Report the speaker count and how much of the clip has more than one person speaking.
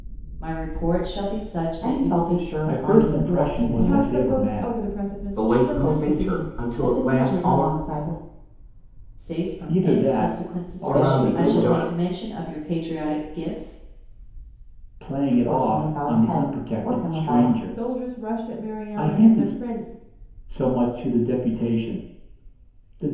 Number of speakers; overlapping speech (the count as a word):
five, about 51%